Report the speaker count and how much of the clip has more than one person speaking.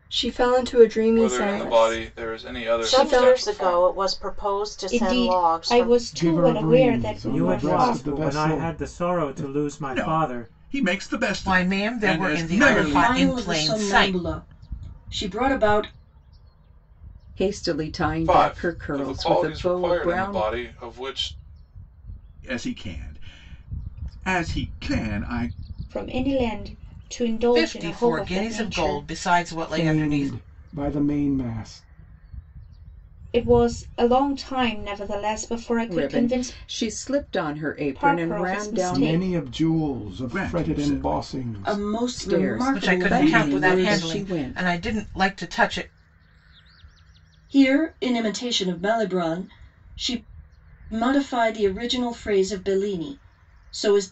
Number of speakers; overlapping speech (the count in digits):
10, about 41%